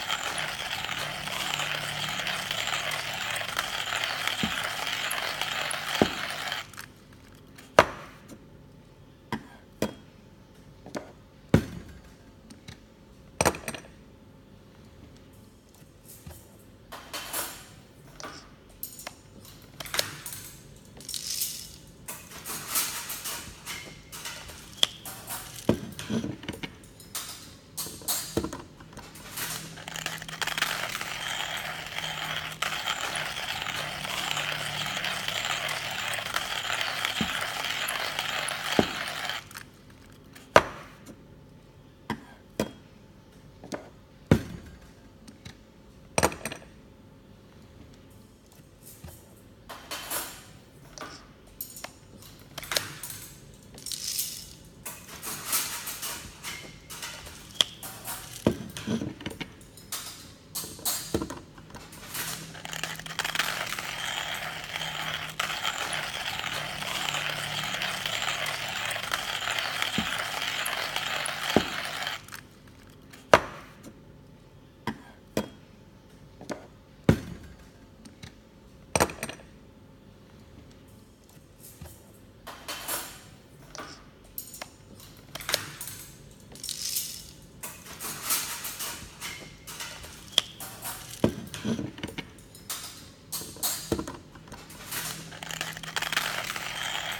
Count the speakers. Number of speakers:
0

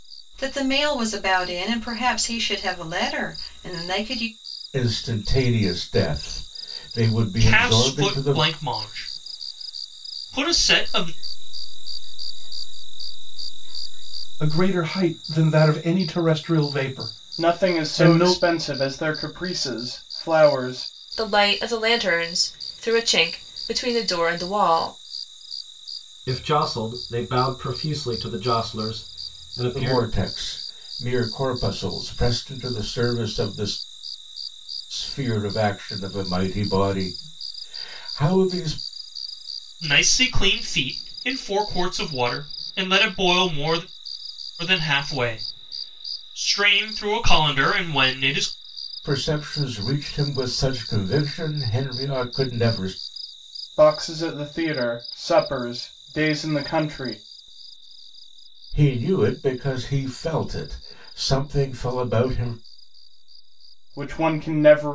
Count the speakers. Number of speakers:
8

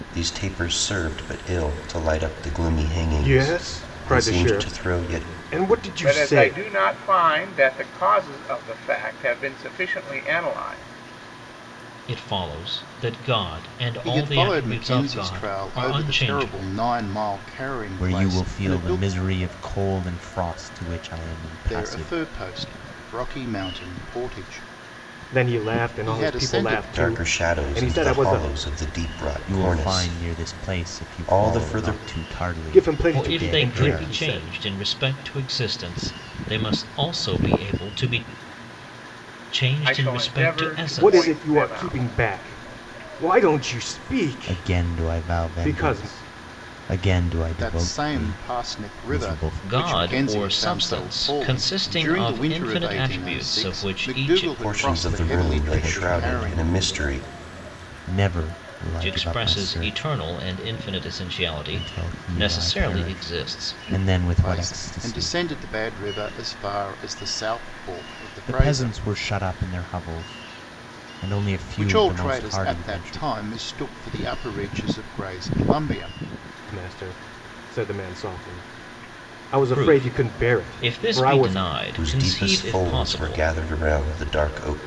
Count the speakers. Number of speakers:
6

